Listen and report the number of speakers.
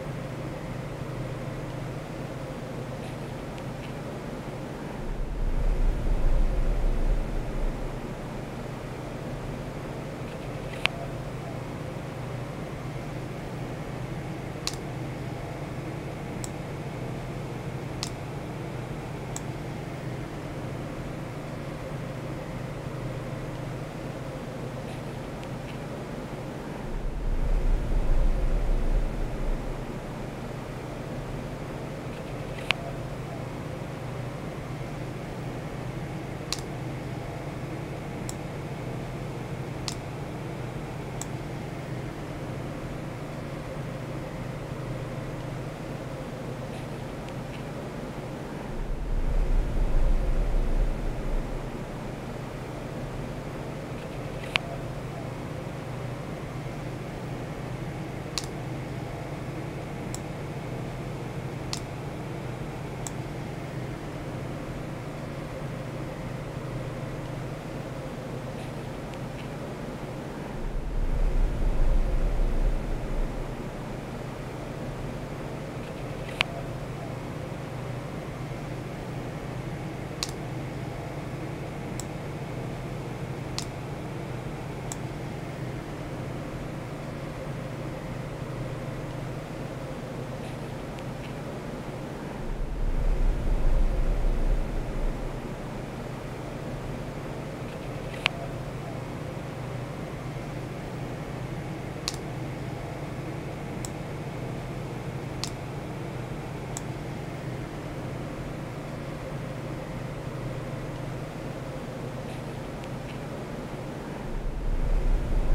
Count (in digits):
0